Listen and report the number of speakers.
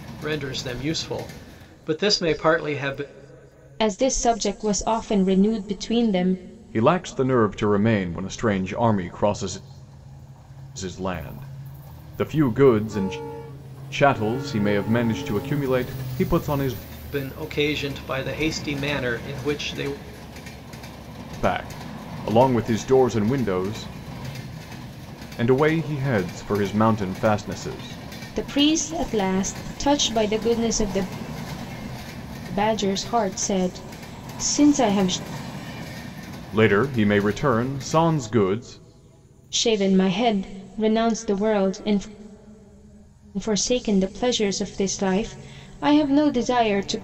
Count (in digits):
3